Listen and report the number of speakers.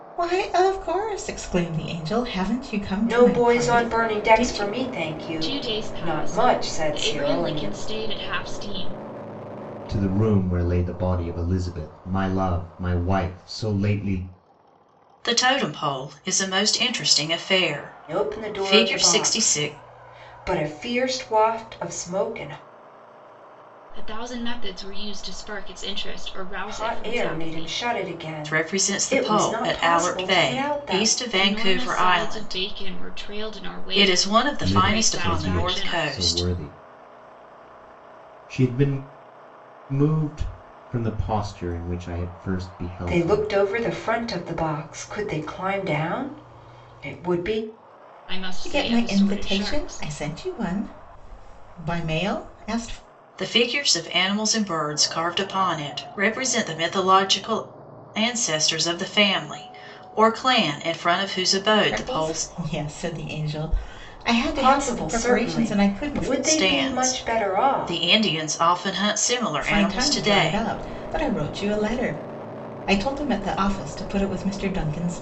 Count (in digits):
5